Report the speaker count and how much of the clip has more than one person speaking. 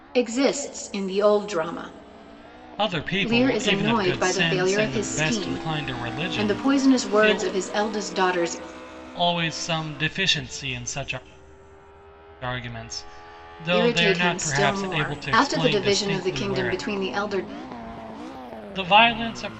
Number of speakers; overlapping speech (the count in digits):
2, about 34%